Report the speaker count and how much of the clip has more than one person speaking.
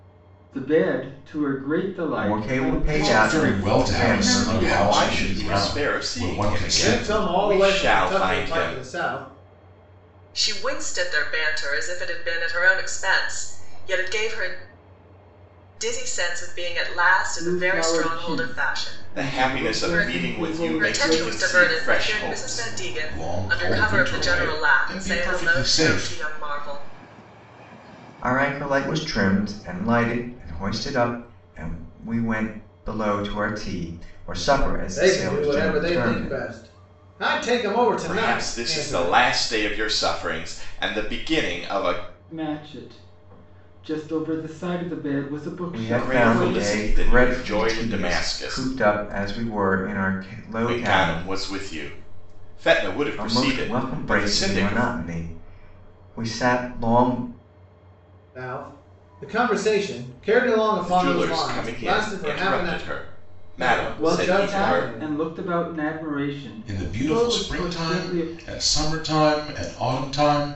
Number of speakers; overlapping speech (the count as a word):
six, about 40%